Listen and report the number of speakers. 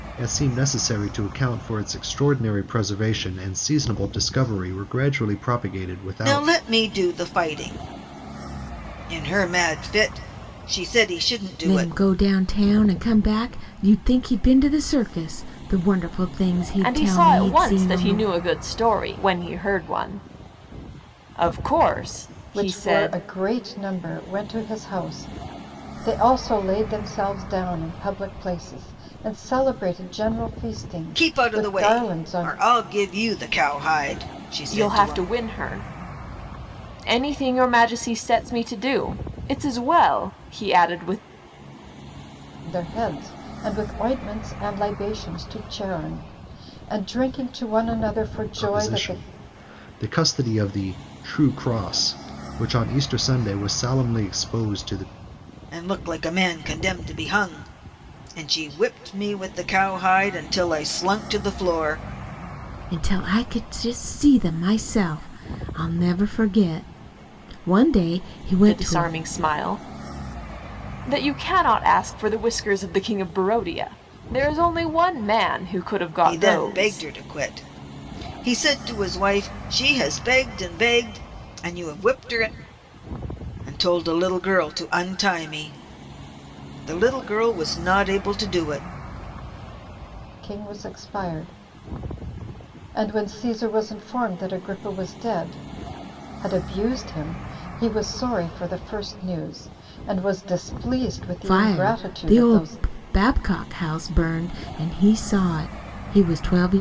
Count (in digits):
5